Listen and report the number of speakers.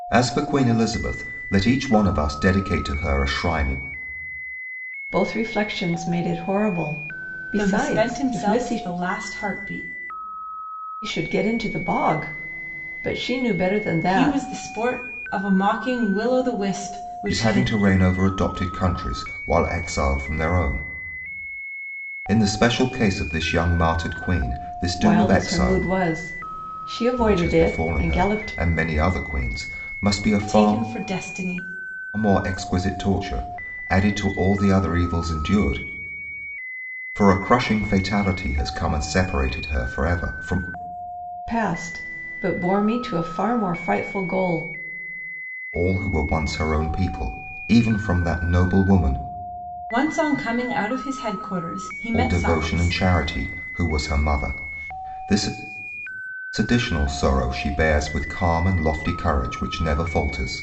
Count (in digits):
3